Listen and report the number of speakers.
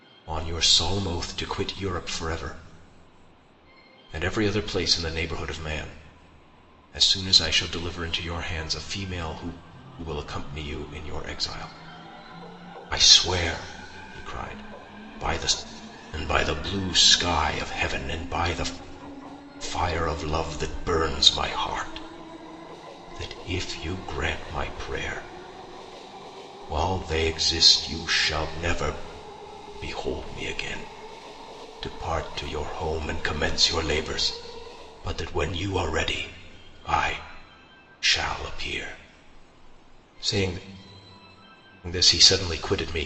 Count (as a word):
one